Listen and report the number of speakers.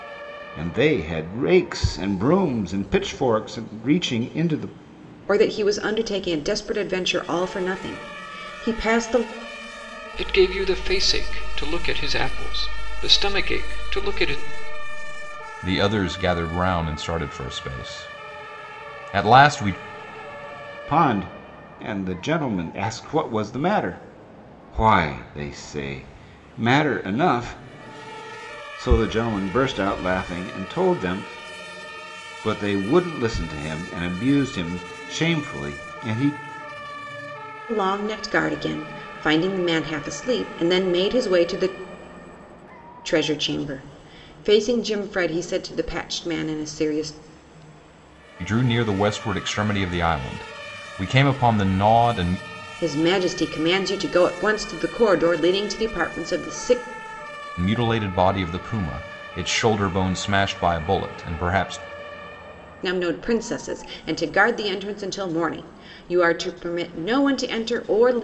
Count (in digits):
4